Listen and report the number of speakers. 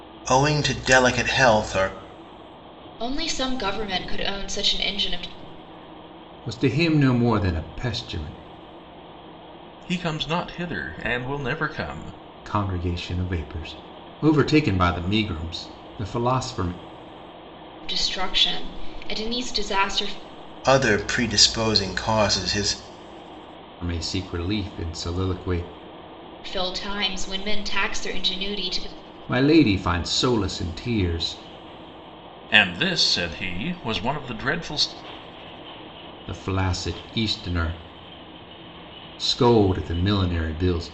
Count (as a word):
four